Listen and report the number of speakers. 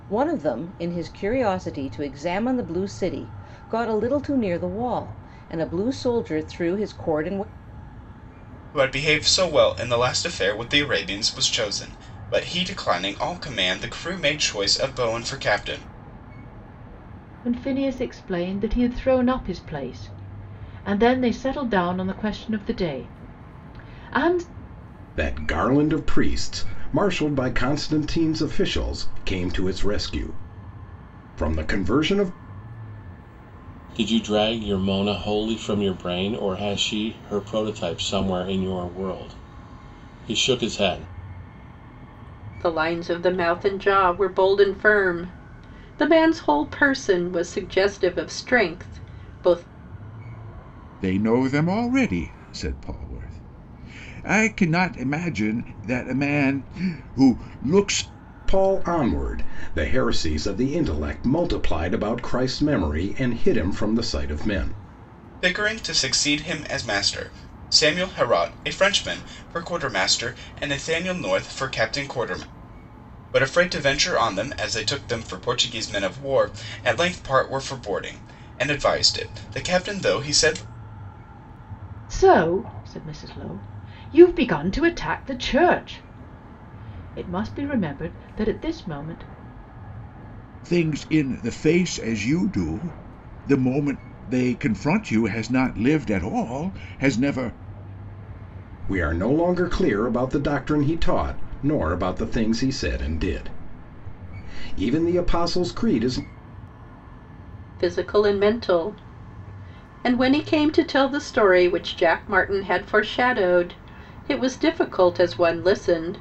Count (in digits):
7